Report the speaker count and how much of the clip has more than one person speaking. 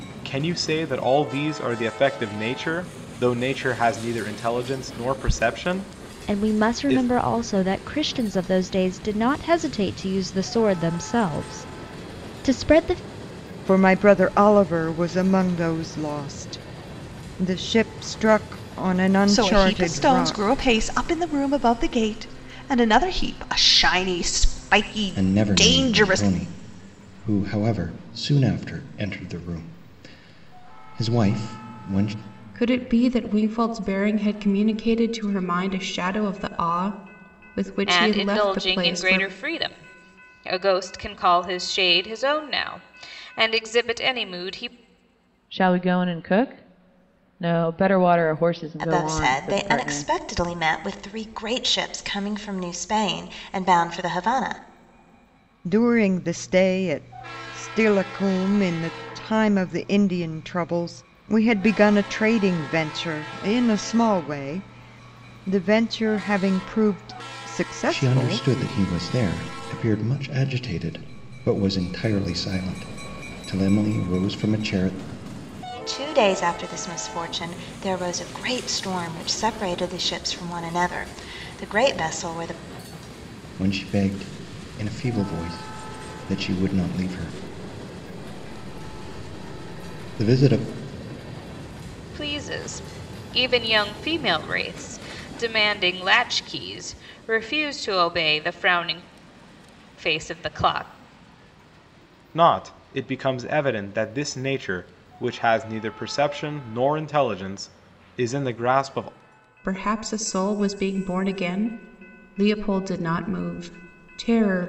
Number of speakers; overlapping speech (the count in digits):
9, about 6%